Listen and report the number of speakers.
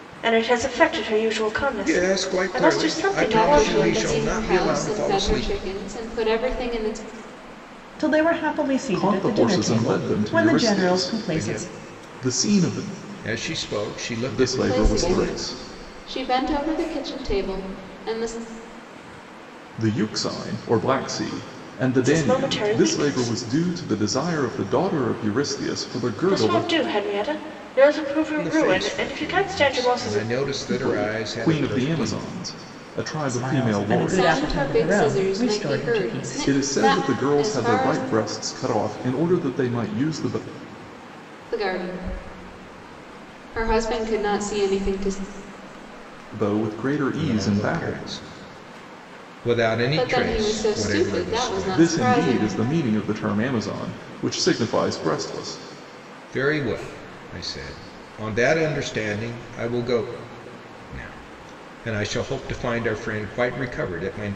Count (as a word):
five